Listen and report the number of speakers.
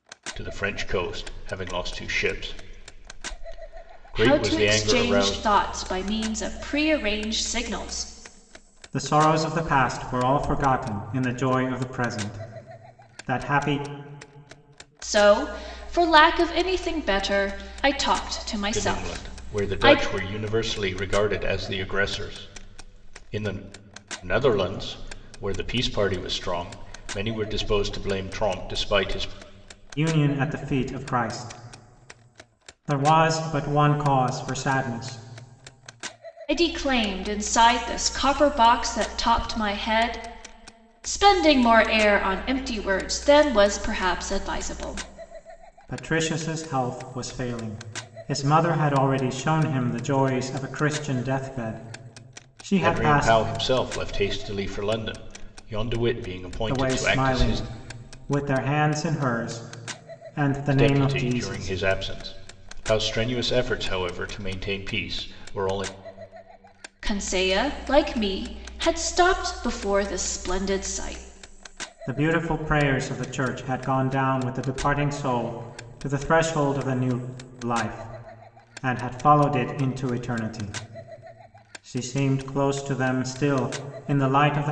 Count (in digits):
3